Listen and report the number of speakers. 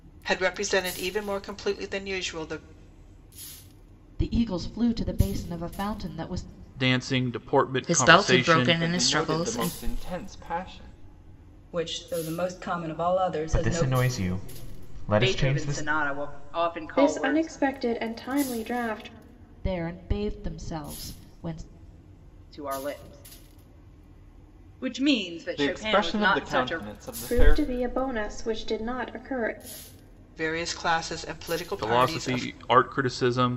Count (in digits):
9